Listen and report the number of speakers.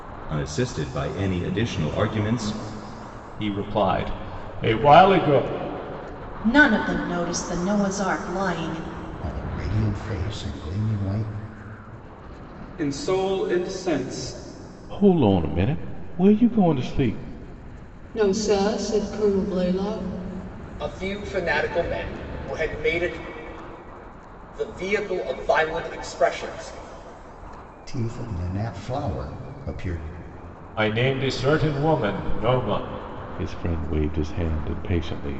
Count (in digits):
8